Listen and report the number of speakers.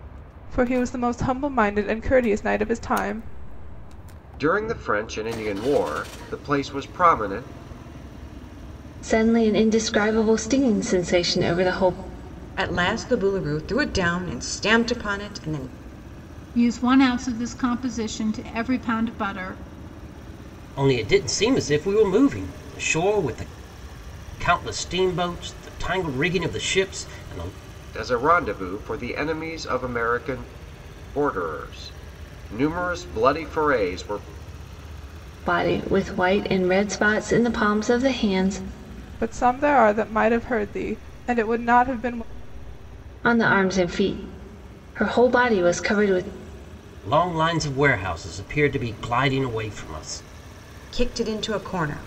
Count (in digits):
6